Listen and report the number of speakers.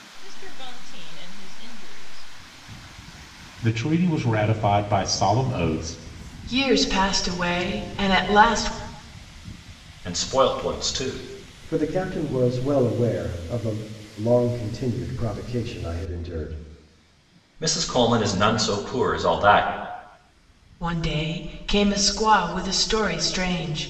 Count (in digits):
5